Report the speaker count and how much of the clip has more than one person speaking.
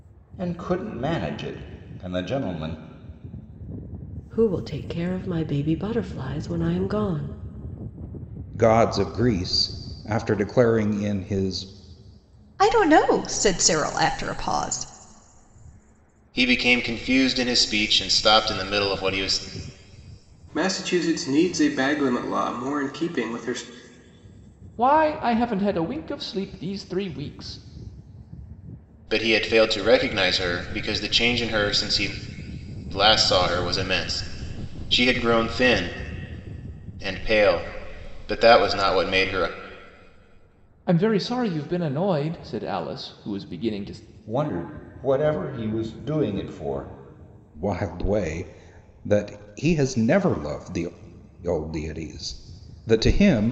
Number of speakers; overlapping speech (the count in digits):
7, no overlap